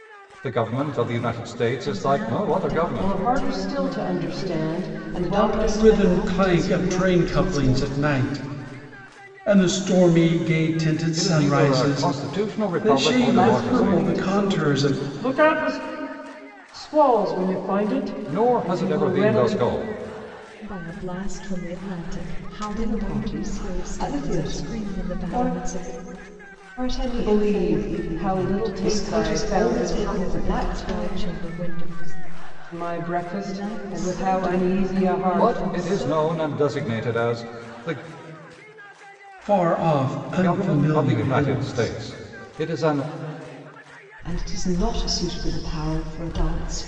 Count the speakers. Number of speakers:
5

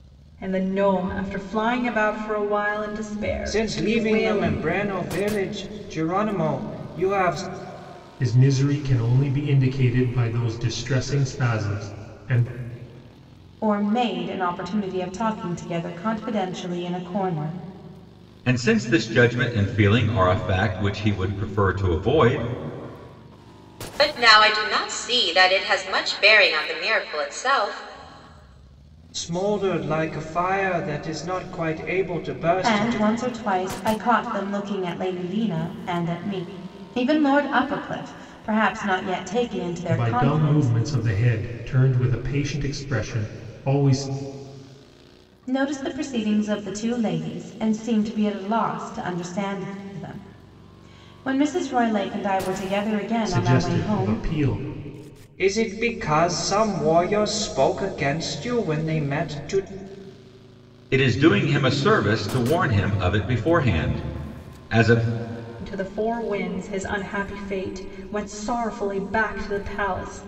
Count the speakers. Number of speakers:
6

